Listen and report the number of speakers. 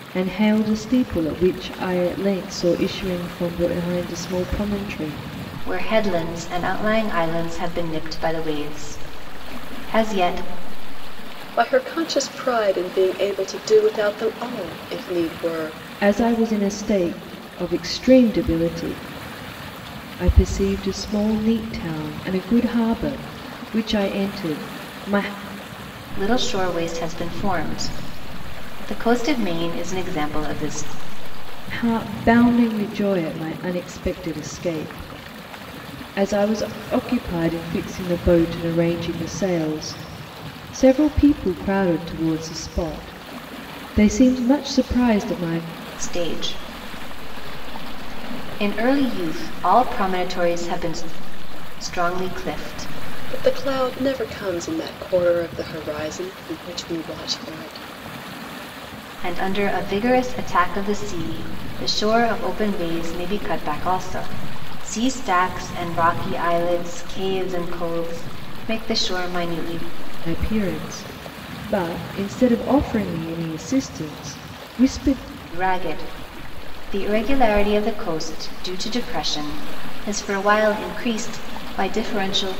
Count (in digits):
3